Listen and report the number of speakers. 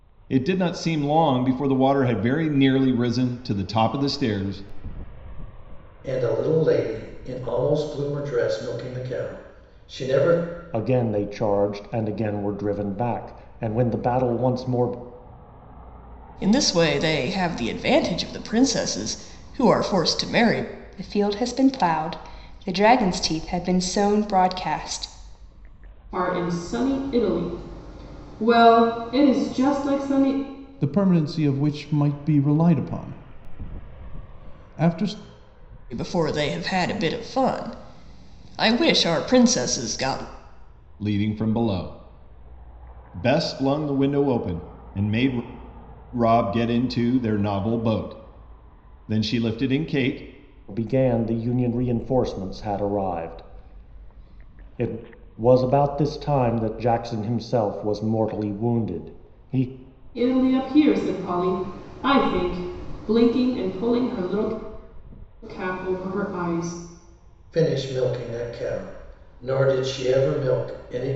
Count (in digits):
7